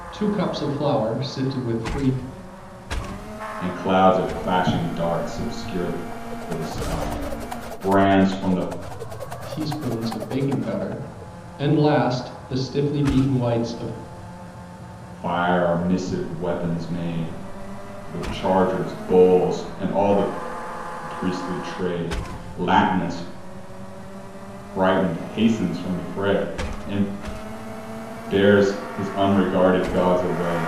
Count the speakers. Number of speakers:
2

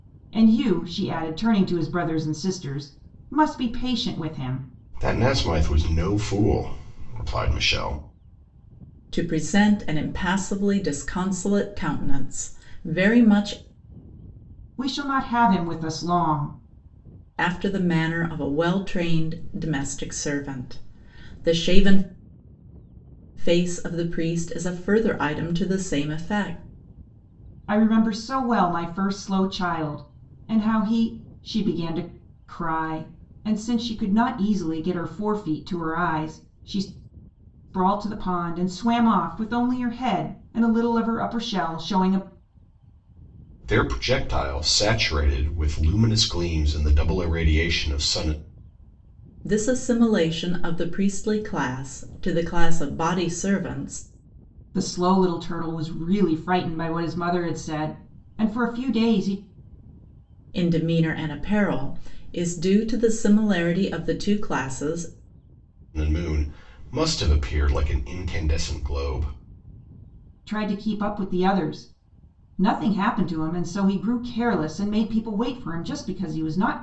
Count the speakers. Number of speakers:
3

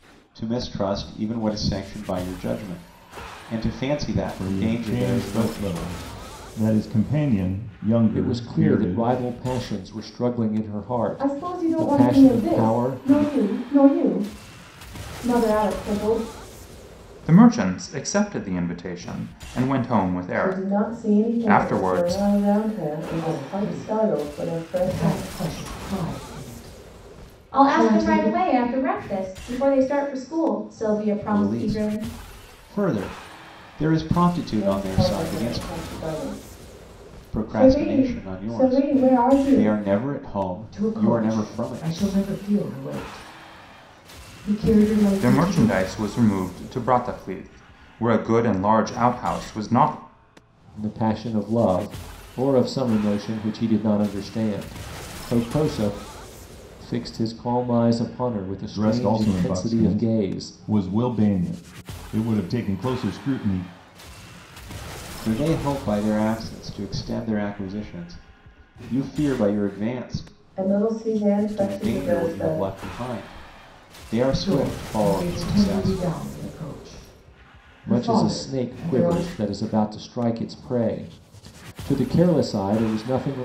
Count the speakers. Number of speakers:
8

